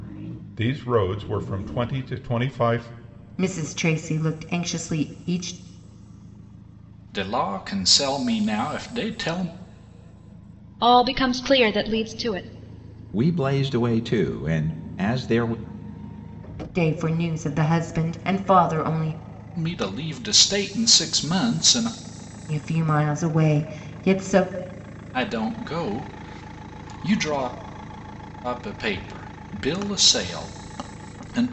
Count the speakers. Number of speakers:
5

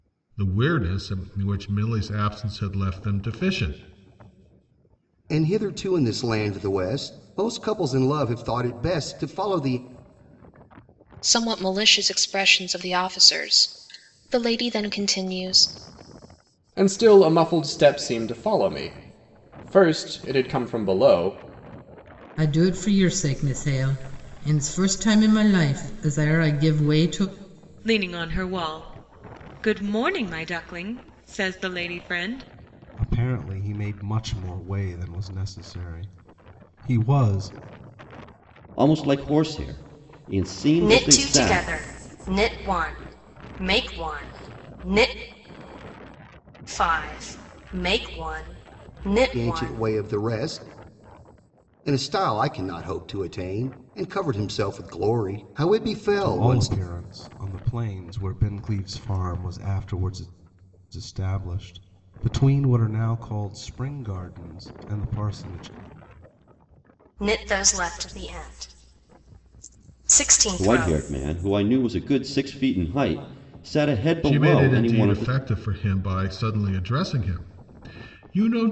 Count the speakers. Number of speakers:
9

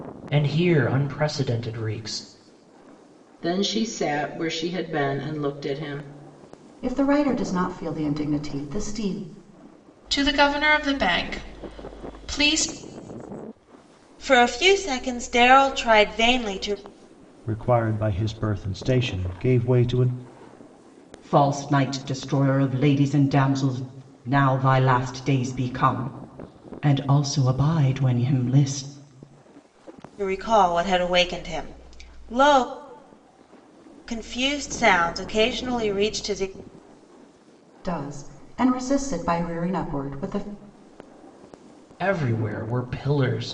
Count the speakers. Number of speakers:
7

